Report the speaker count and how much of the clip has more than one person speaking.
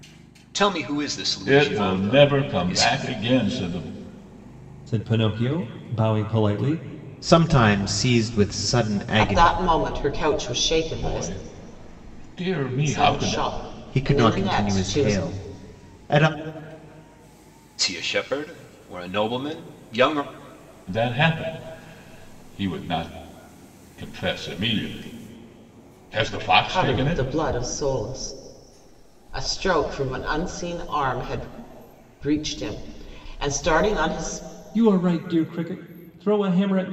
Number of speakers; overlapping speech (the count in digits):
5, about 13%